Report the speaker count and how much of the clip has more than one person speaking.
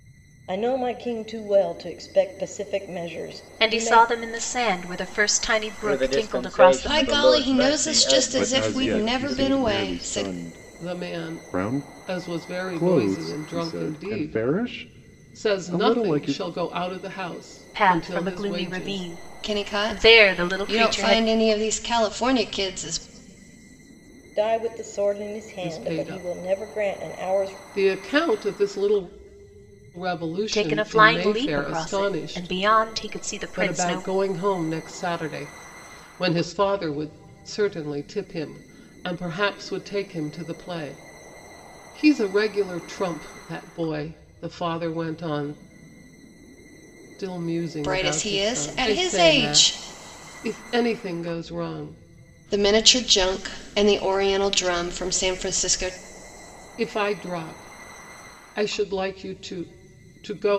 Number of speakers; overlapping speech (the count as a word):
six, about 31%